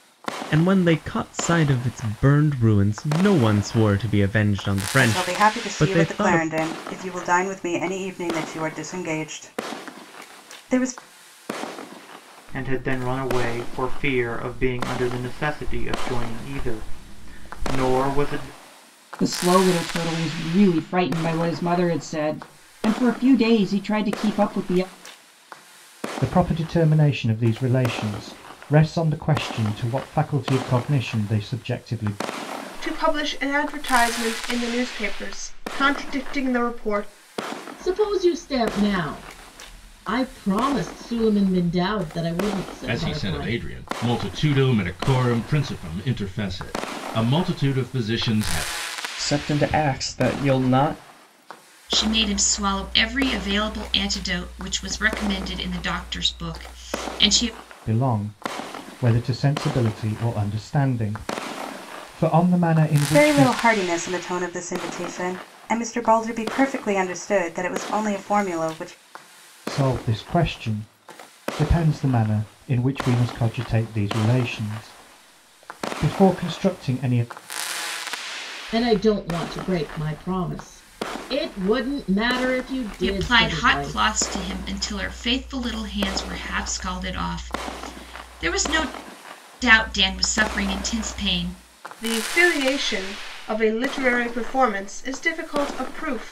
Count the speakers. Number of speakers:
10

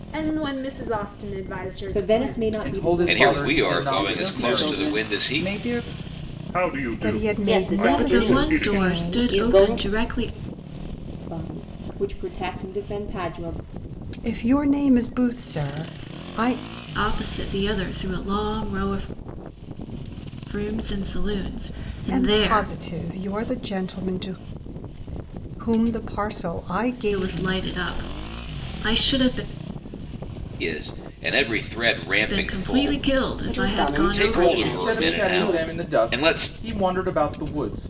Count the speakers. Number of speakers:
9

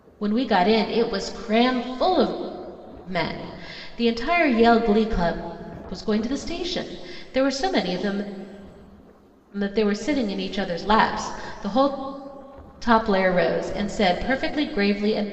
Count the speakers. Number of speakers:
1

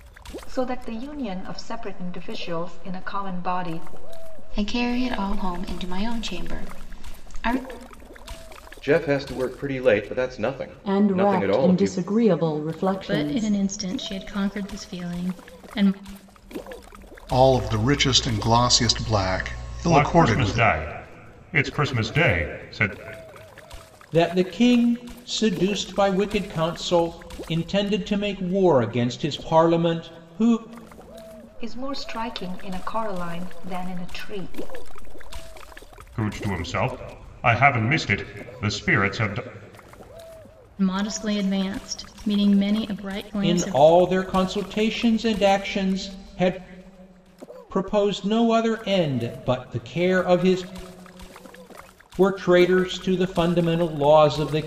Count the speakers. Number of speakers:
8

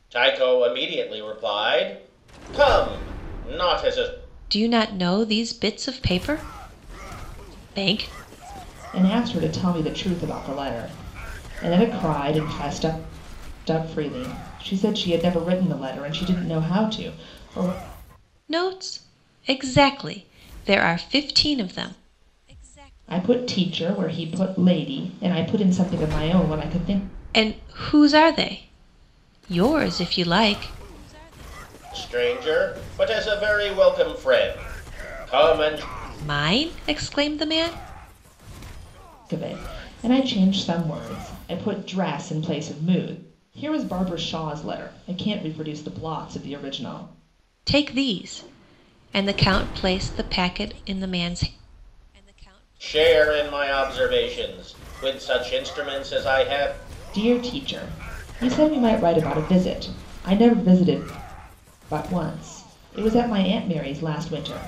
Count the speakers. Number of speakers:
3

